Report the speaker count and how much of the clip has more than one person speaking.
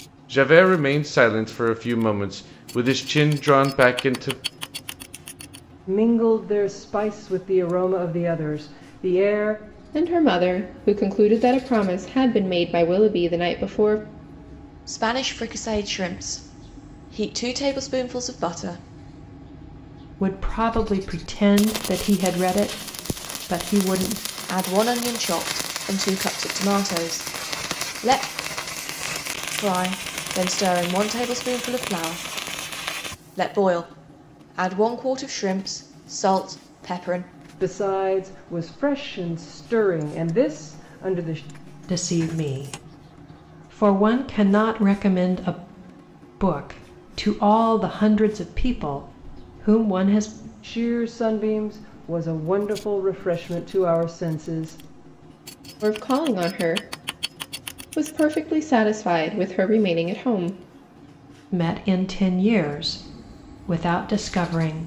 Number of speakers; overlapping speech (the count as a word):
five, no overlap